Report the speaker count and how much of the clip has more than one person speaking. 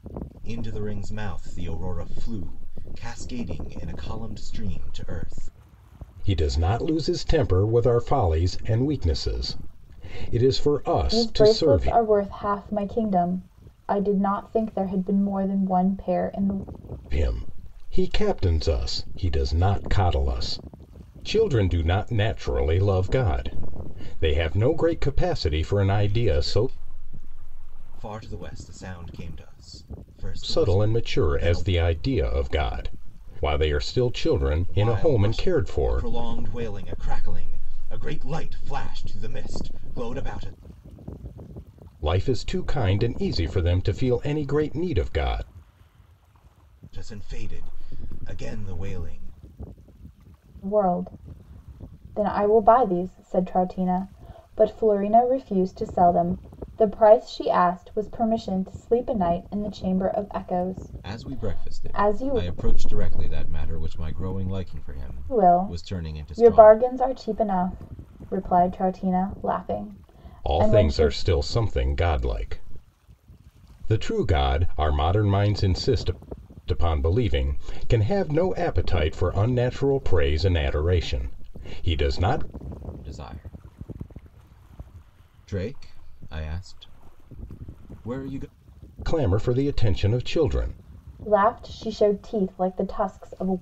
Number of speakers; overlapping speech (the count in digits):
3, about 8%